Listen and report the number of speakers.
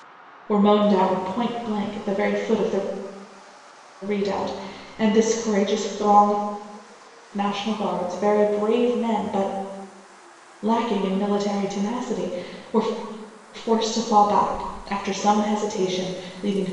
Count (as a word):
one